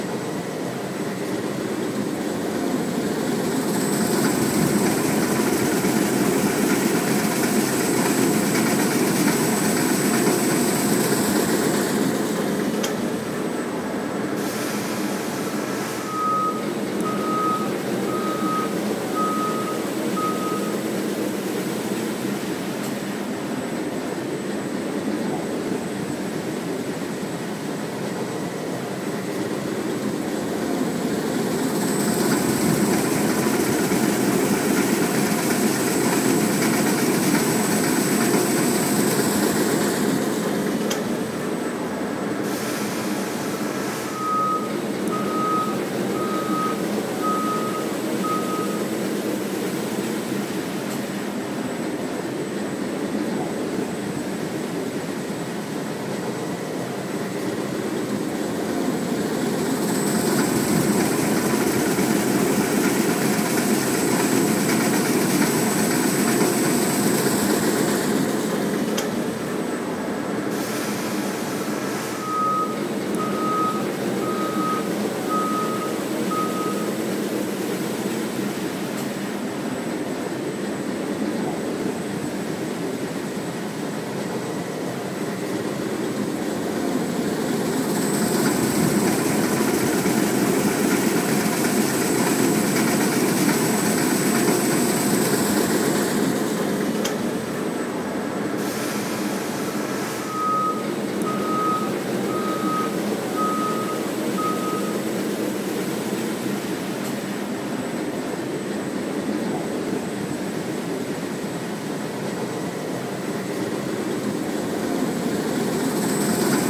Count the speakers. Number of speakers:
zero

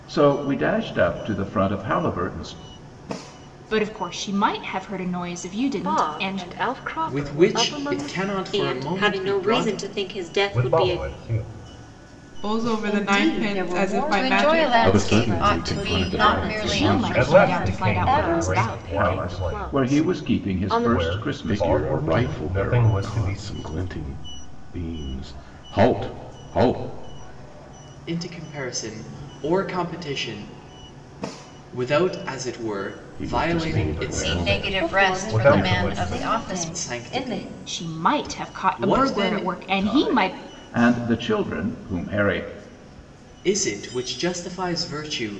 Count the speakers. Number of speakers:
ten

